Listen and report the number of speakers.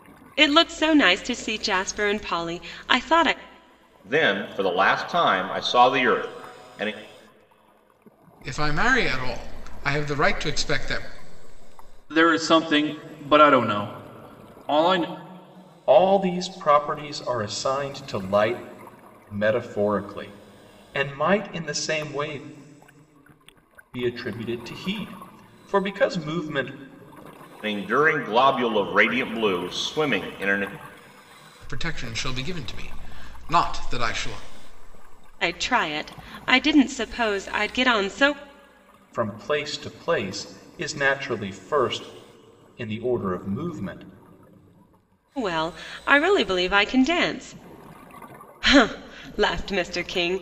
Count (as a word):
five